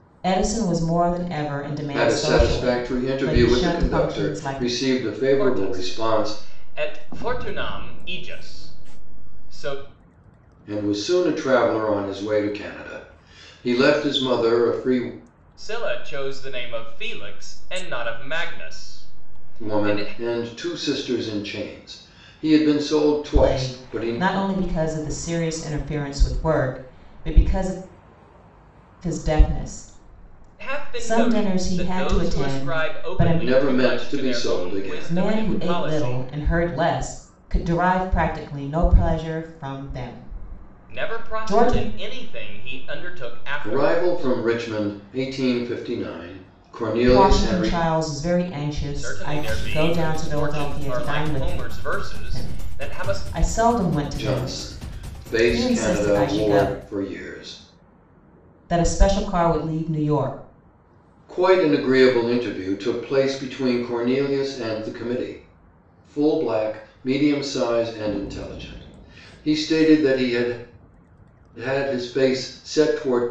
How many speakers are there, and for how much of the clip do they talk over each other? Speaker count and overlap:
3, about 27%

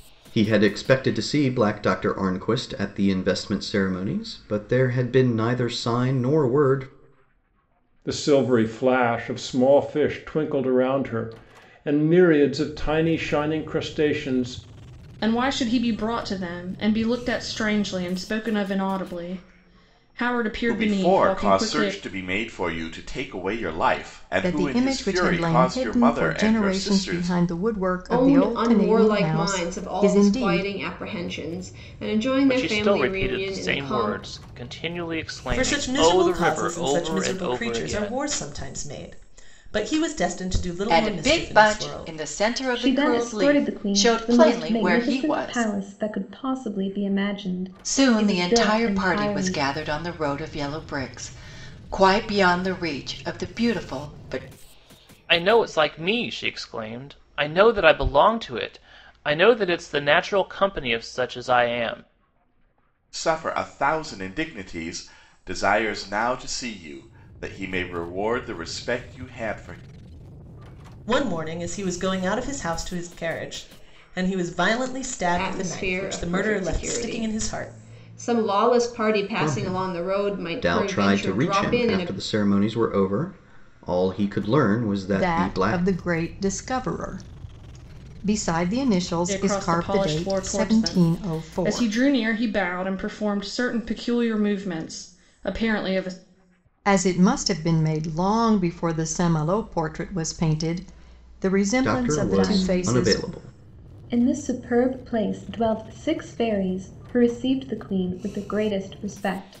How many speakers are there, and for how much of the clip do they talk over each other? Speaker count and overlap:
10, about 26%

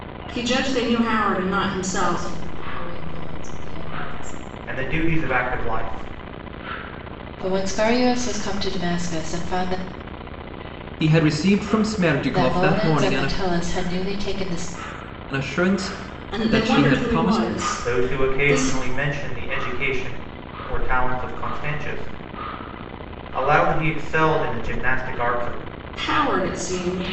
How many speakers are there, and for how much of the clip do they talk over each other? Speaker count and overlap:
5, about 14%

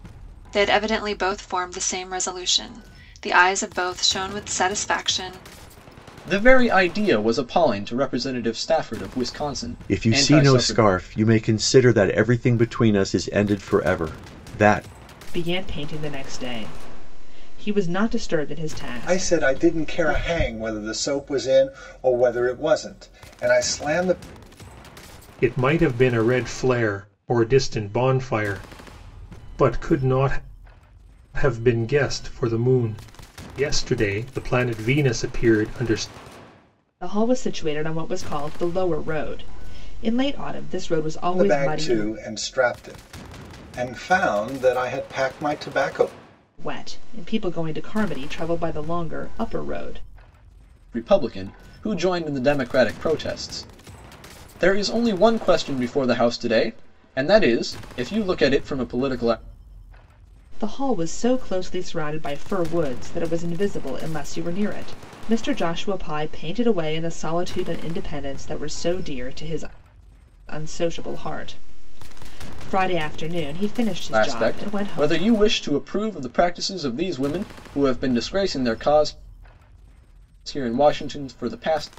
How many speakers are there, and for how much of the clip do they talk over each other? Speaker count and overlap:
6, about 5%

